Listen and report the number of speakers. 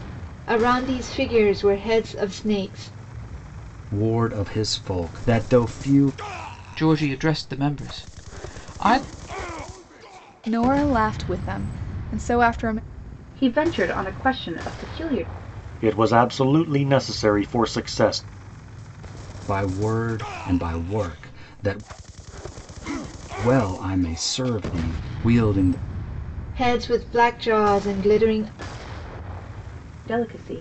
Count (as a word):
six